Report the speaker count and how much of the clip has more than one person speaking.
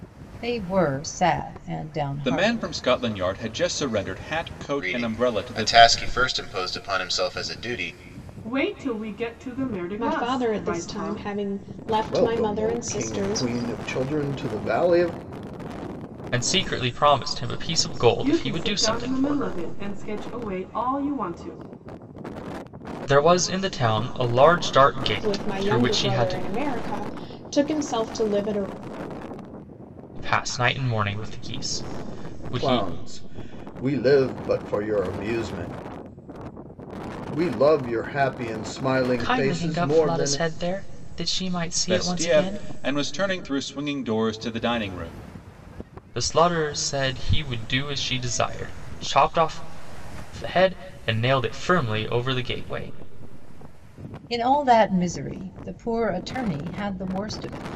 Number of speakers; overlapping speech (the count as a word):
seven, about 16%